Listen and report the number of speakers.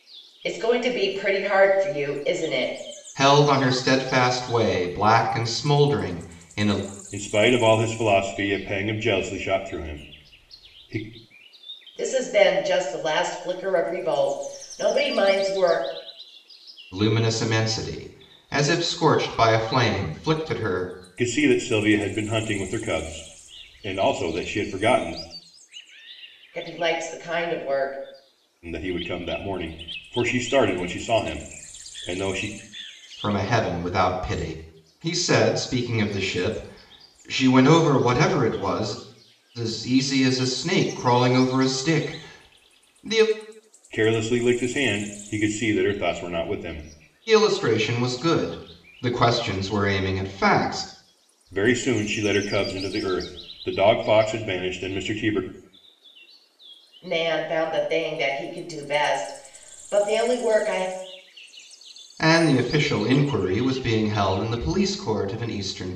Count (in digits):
3